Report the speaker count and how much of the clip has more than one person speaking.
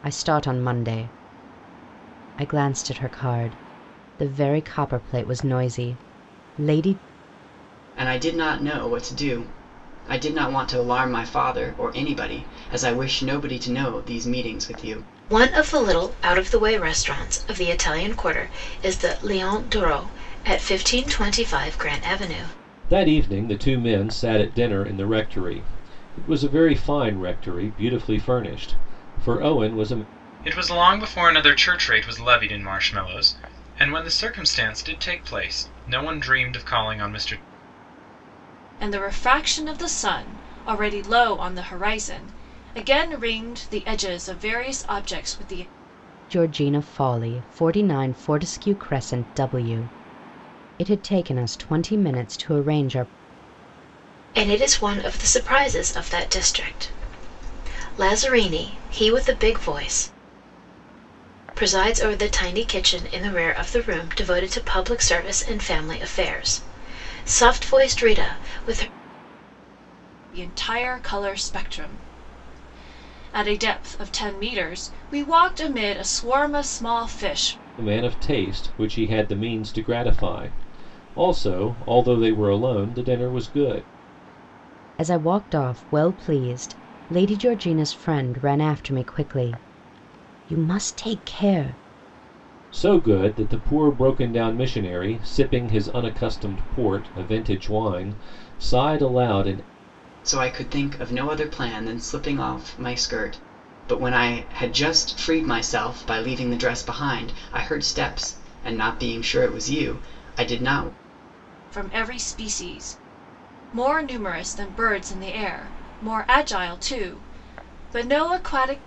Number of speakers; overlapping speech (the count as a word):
six, no overlap